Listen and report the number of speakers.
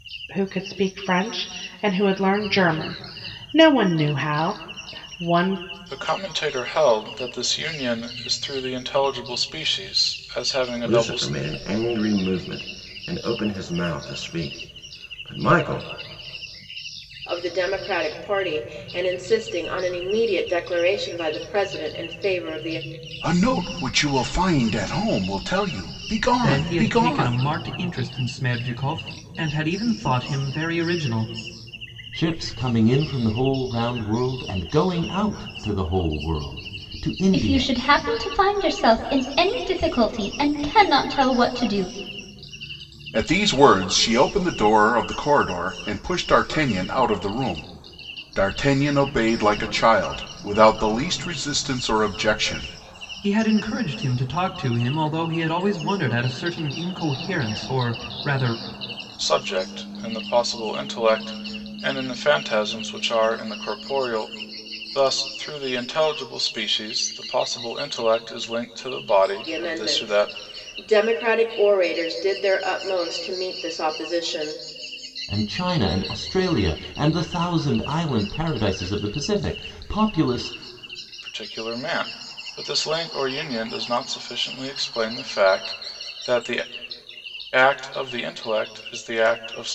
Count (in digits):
8